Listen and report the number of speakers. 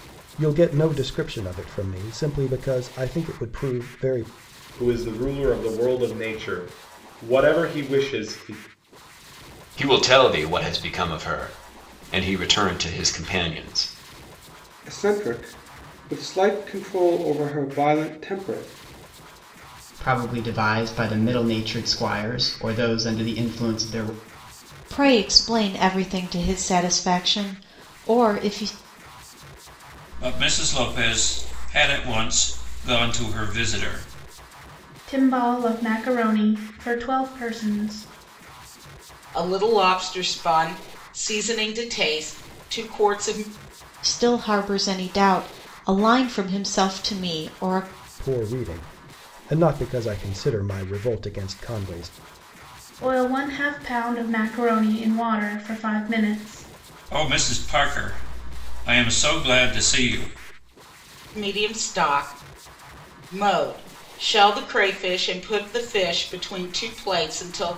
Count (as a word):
nine